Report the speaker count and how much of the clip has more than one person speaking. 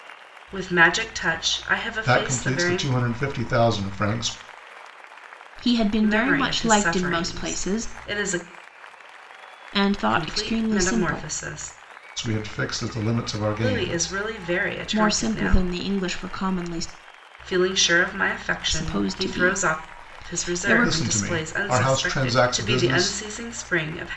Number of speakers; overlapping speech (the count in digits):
3, about 39%